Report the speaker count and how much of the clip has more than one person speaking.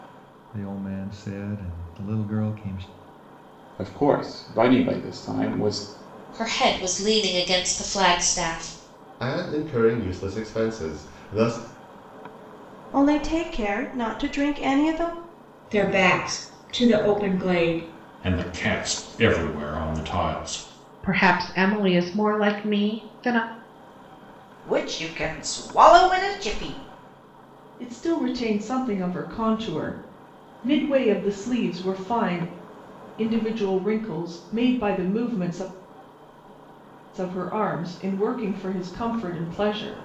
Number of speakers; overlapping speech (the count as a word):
ten, no overlap